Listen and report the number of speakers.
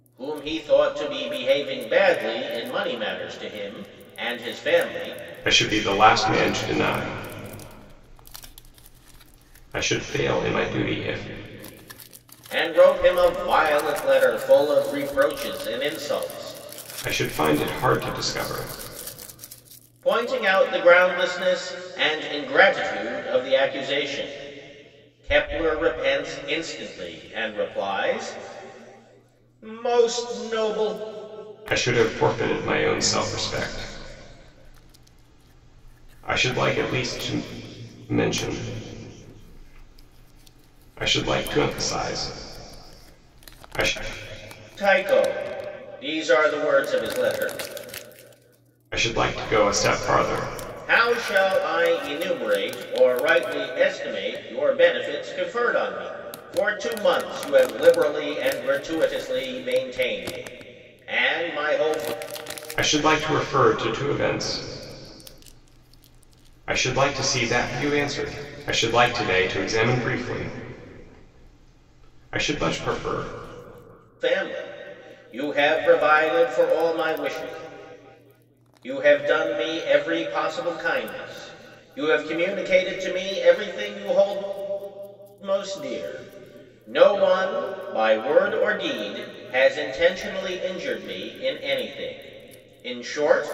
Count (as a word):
two